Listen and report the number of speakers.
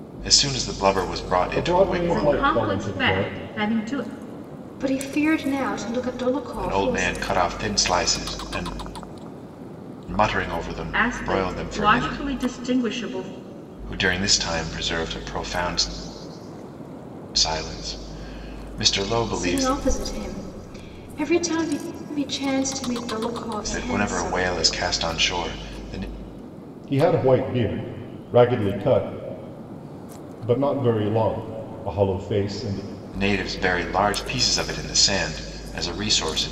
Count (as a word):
four